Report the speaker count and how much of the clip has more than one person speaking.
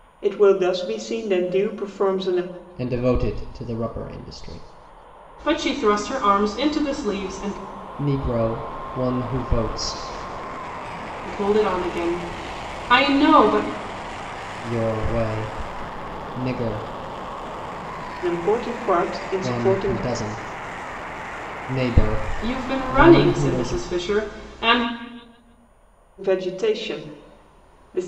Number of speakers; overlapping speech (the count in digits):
3, about 7%